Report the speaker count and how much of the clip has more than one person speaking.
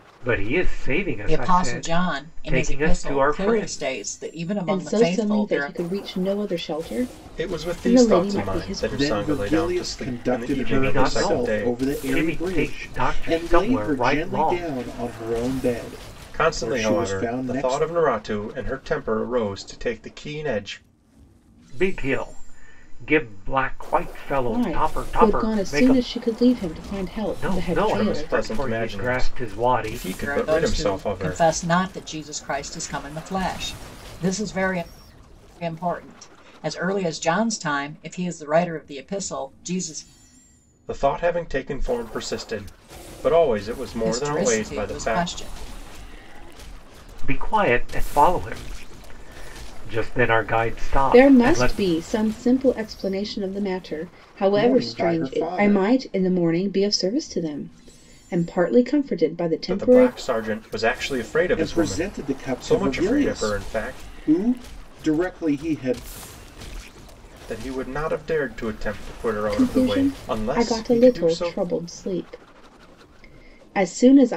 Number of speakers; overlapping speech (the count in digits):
5, about 36%